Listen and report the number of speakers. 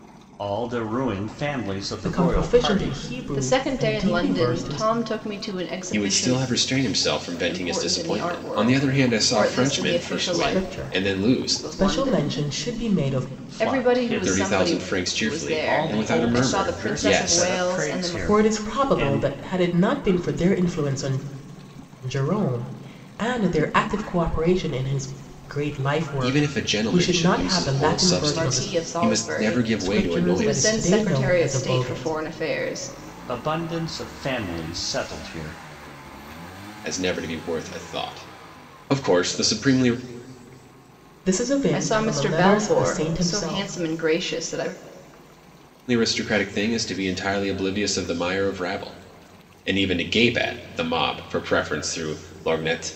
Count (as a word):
four